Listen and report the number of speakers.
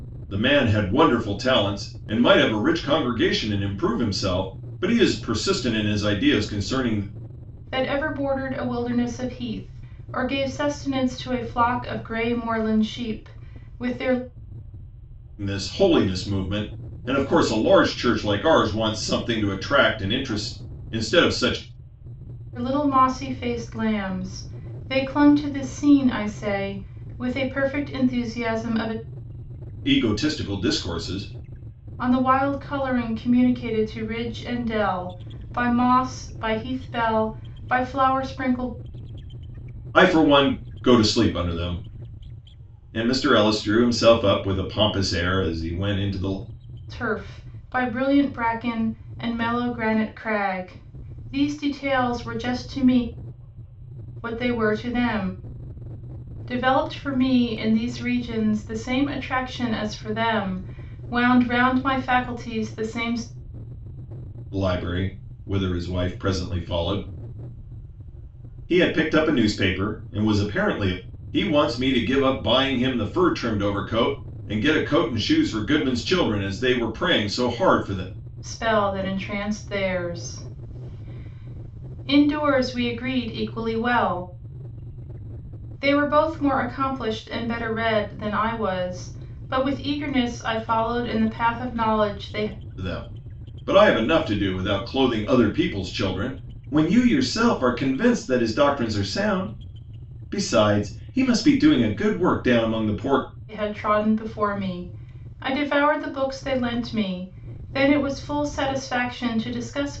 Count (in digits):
2